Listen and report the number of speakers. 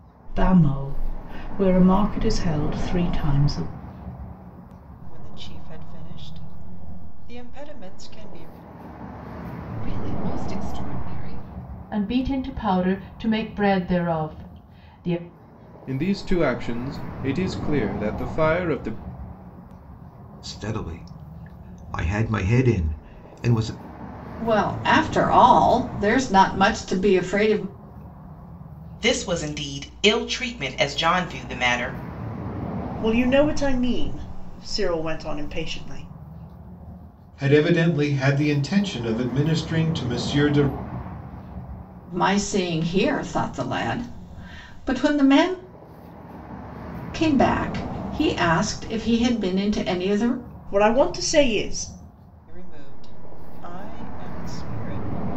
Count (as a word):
ten